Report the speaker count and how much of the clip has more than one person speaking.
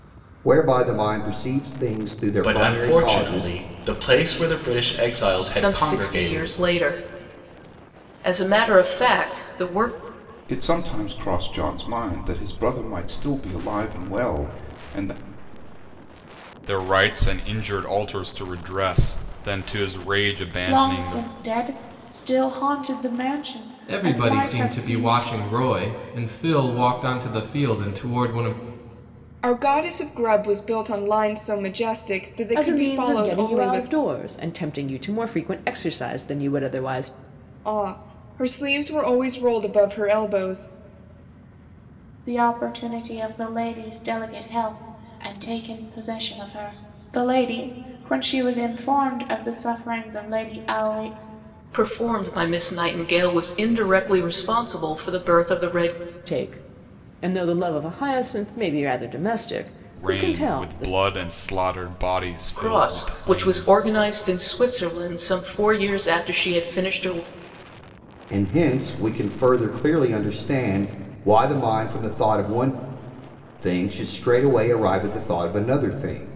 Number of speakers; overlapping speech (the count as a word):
nine, about 10%